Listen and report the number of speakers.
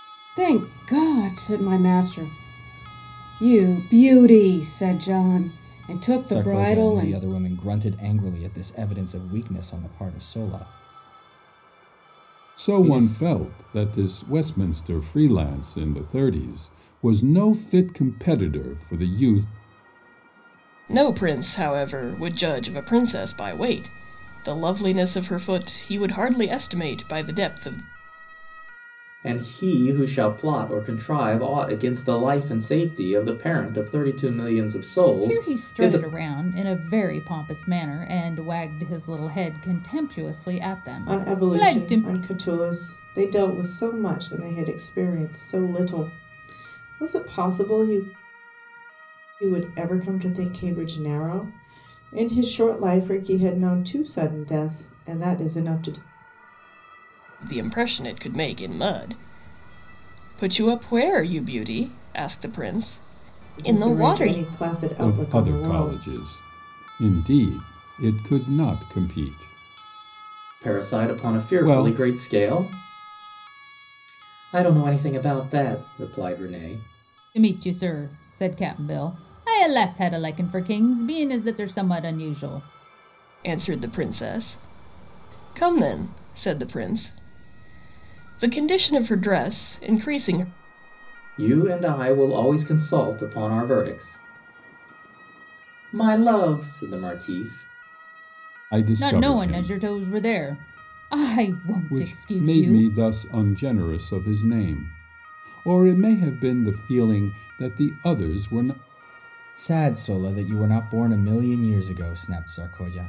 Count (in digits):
7